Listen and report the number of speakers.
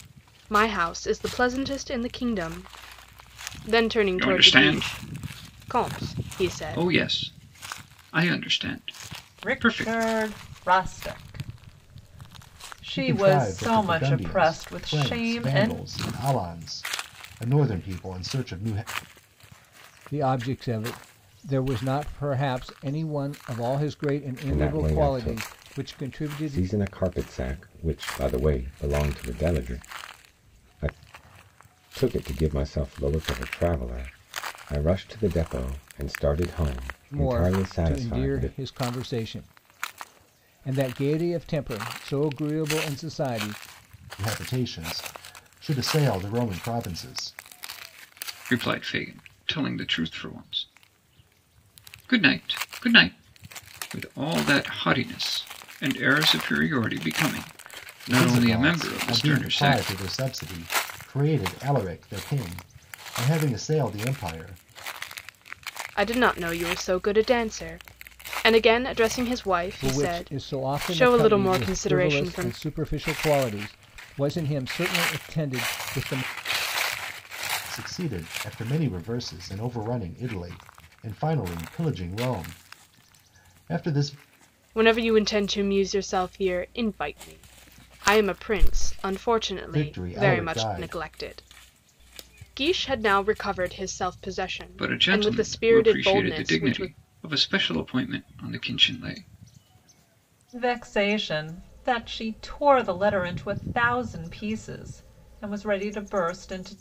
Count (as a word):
six